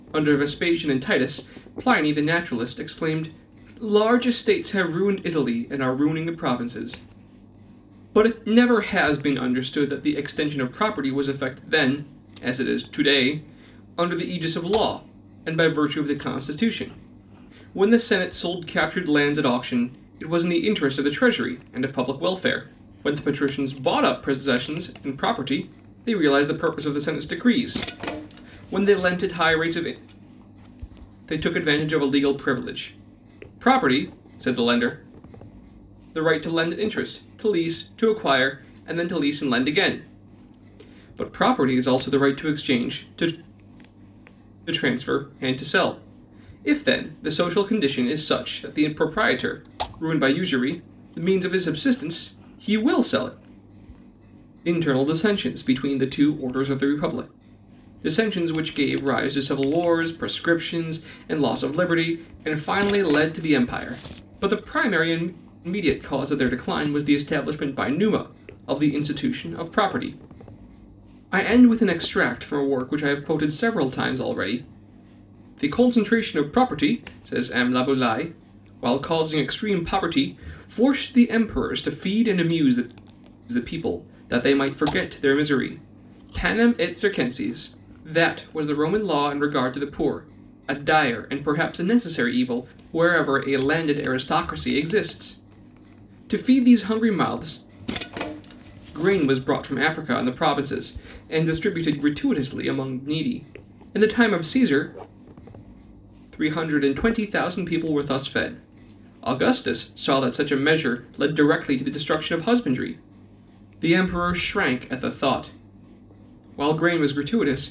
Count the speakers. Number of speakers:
1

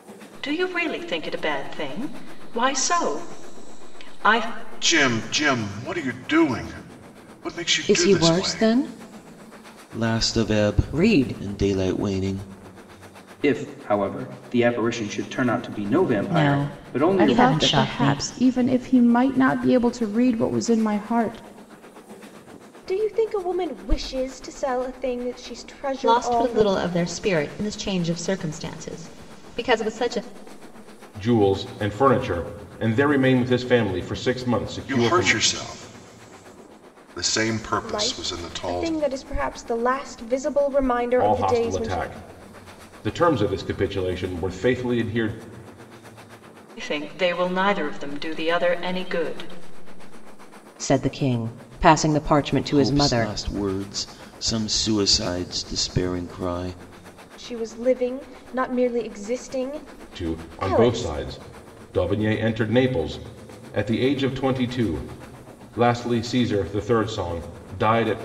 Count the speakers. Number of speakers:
10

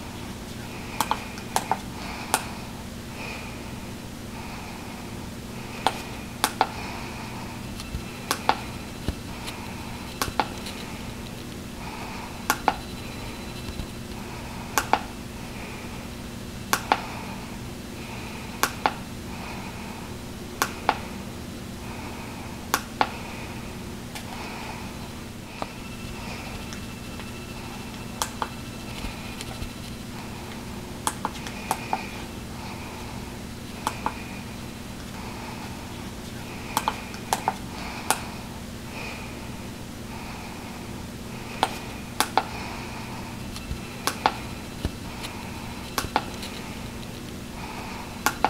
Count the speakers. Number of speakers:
0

